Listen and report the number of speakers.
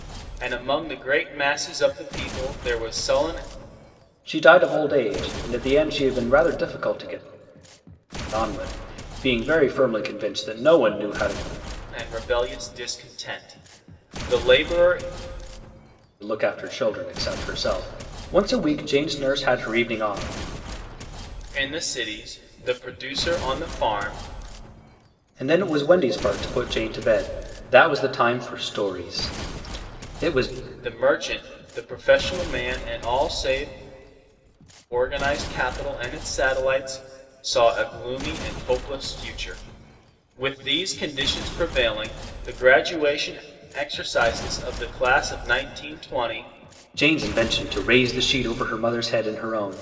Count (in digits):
2